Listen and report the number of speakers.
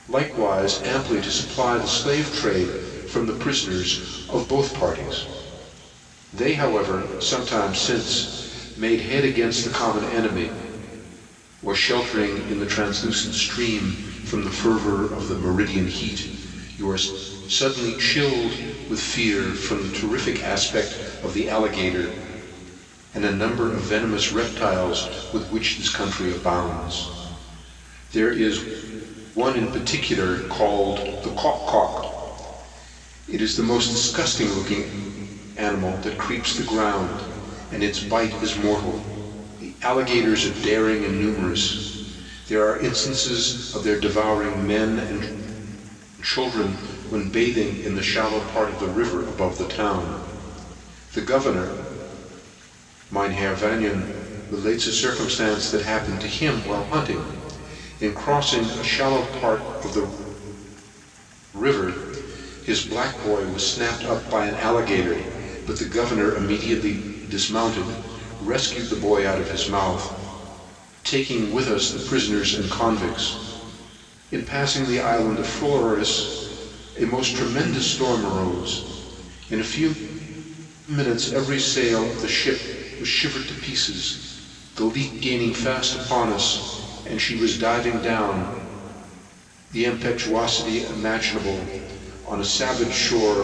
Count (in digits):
1